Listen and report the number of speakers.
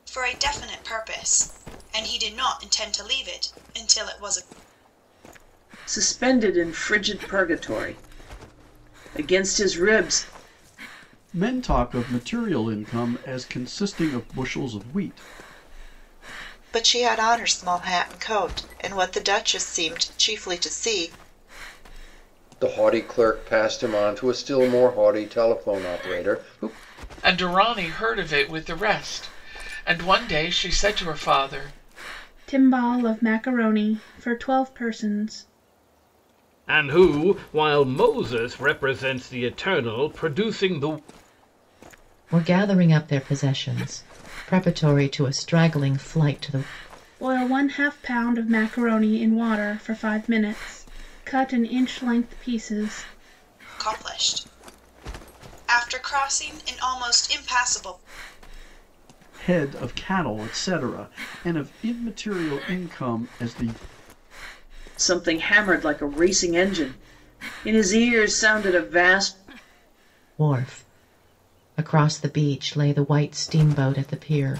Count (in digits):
9